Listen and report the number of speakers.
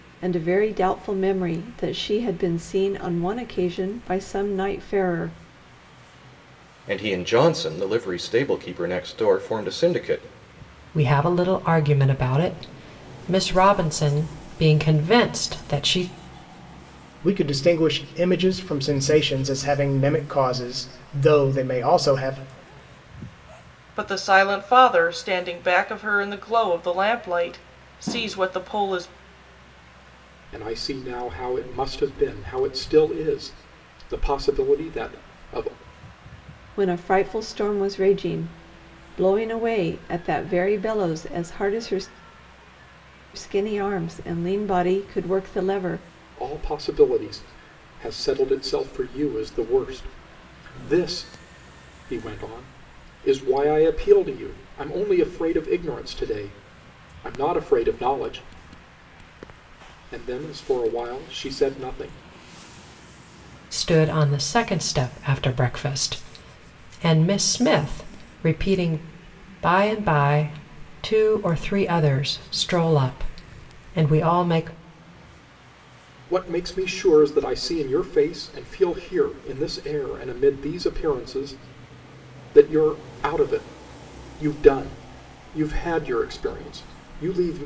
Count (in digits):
6